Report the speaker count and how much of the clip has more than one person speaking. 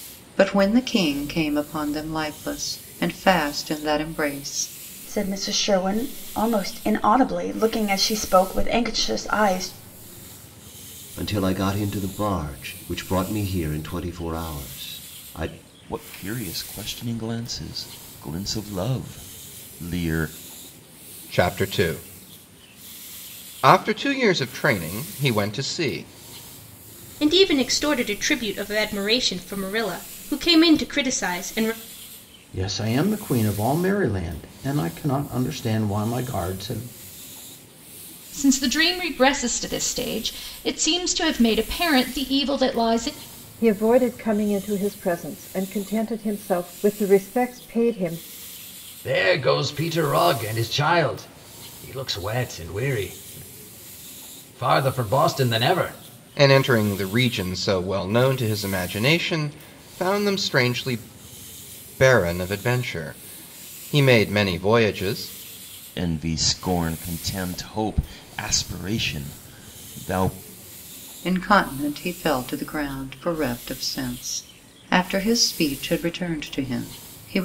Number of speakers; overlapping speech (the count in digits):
10, no overlap